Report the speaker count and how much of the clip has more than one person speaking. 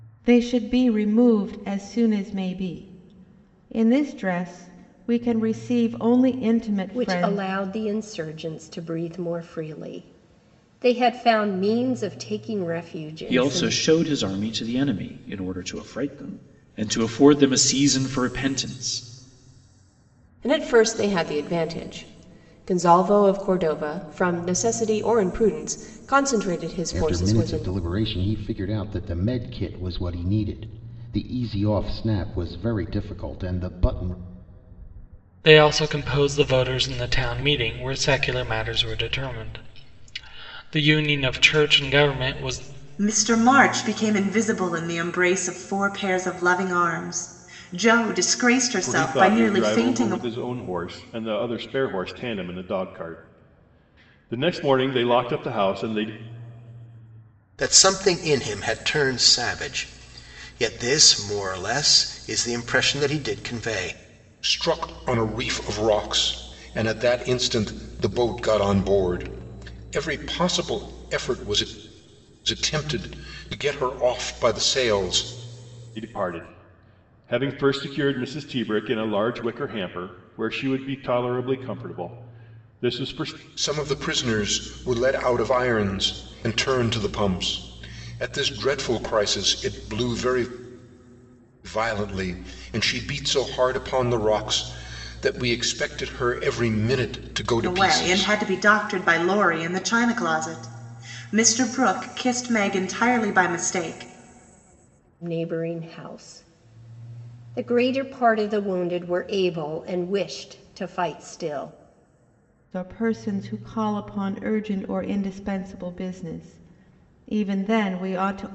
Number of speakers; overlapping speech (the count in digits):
10, about 4%